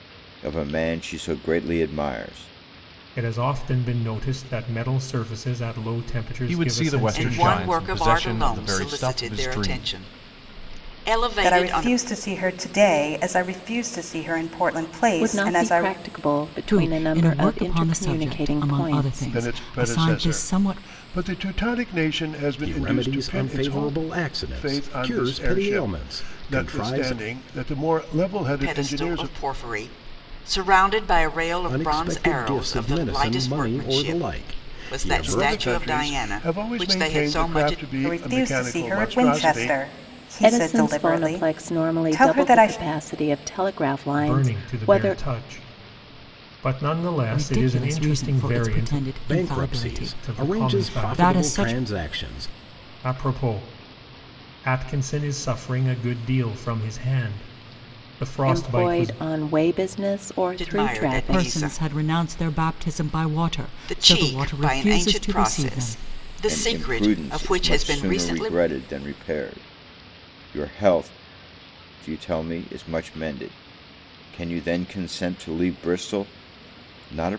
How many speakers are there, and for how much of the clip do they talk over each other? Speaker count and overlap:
nine, about 48%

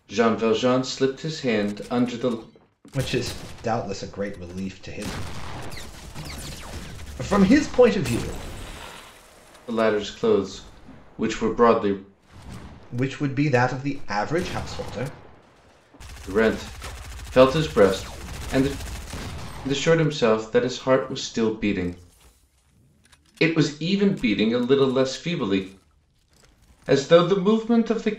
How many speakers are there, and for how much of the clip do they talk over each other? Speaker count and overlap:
two, no overlap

